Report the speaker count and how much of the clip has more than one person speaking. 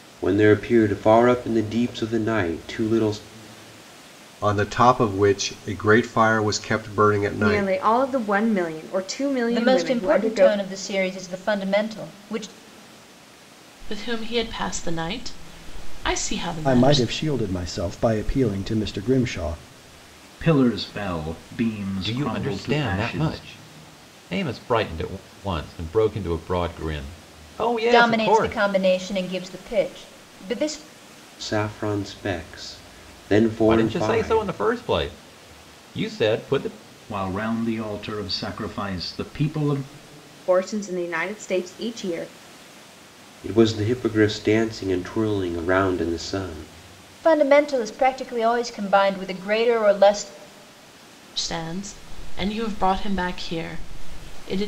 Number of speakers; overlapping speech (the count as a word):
eight, about 9%